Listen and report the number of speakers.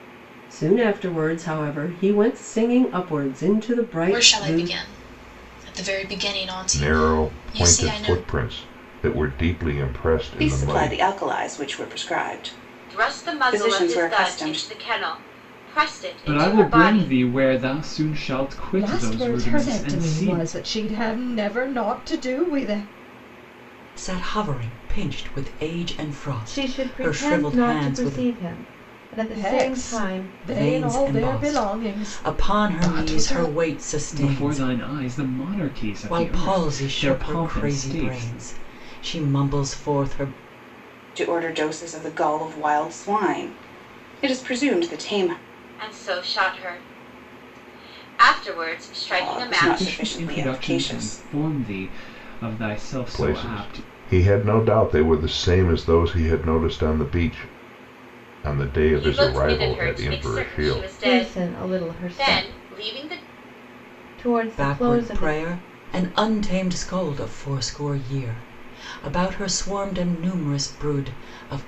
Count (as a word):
nine